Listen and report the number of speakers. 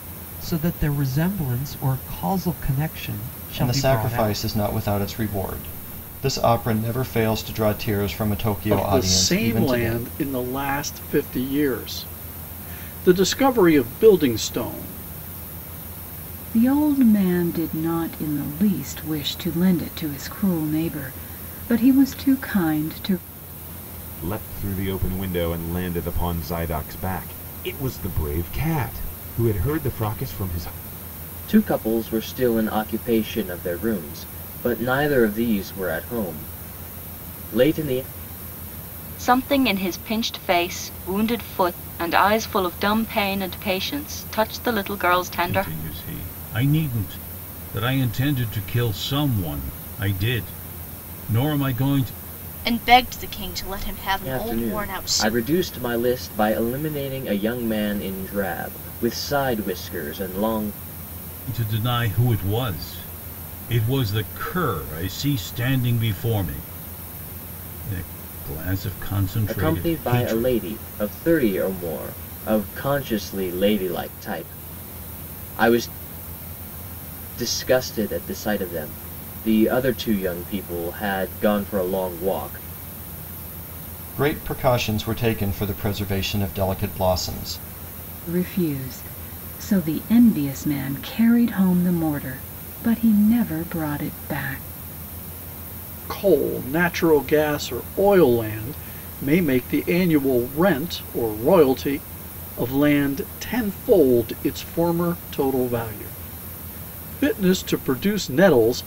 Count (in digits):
9